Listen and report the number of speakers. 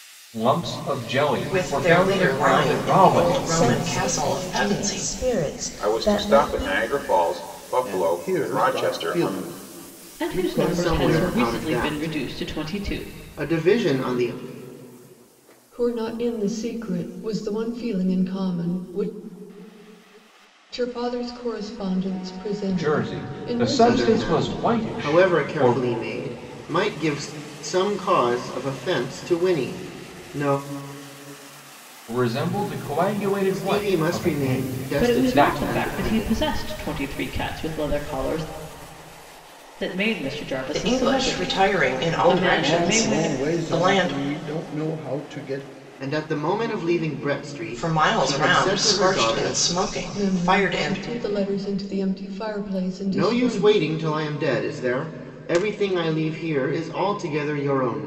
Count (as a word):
eight